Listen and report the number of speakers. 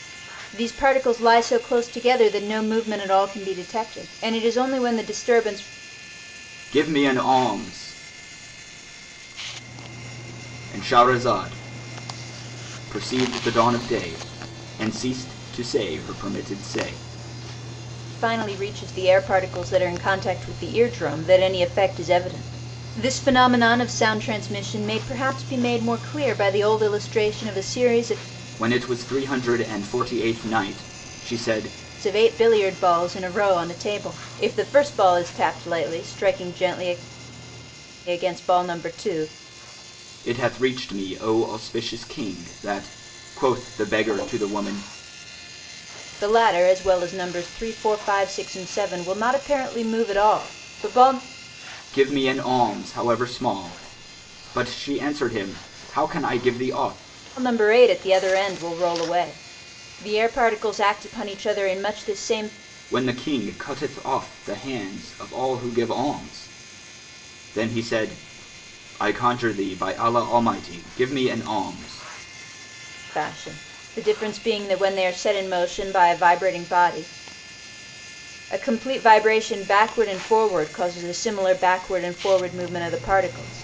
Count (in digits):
2